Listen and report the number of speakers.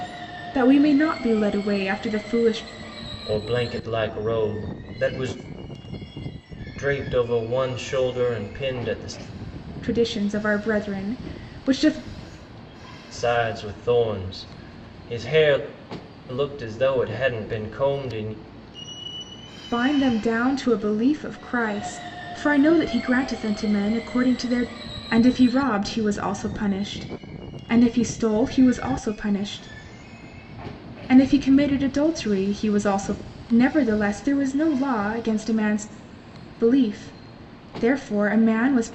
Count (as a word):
two